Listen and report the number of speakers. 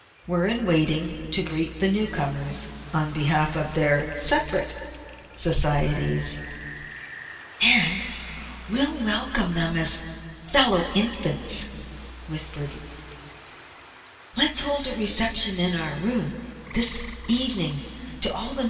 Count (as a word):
one